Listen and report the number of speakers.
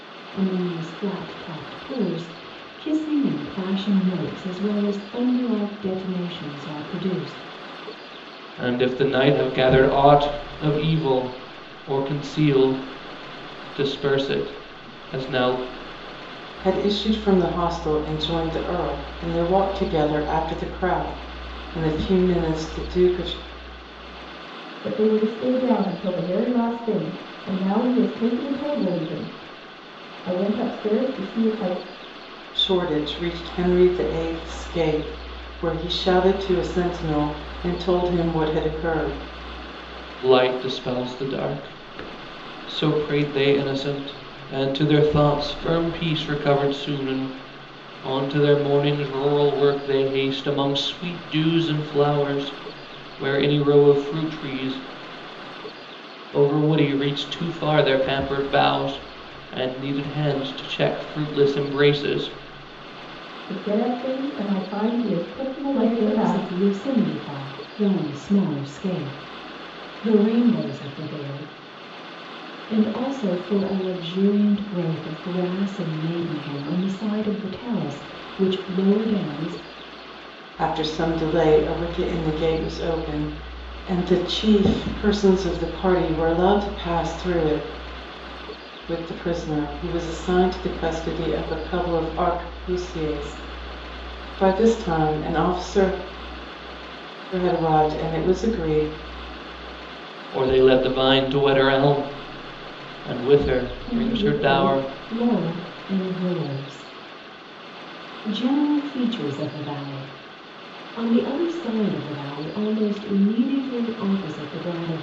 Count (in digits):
4